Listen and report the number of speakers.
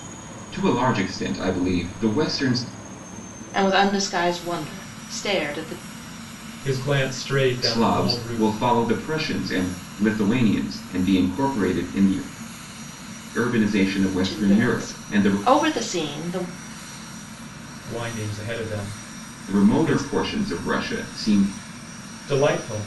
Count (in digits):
3